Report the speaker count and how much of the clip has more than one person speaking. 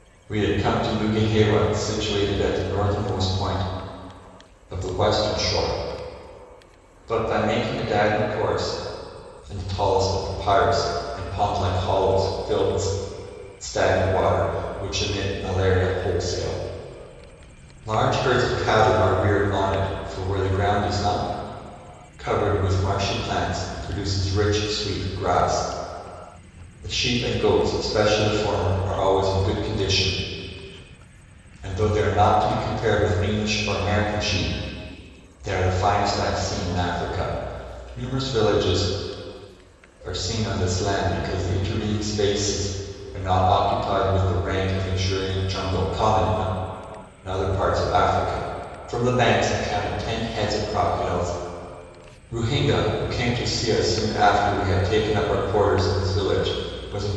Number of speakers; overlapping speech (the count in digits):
1, no overlap